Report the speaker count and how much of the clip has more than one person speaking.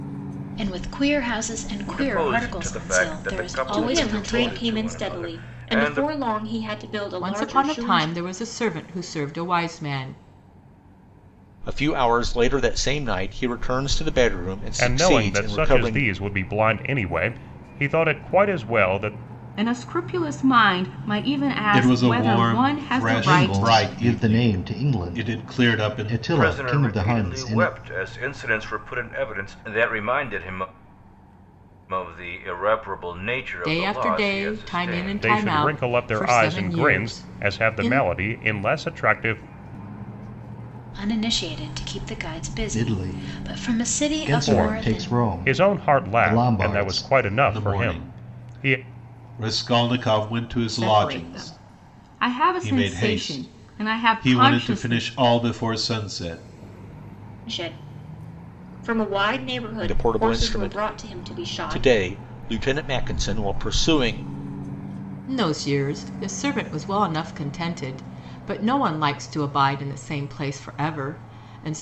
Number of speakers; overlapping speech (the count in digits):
9, about 39%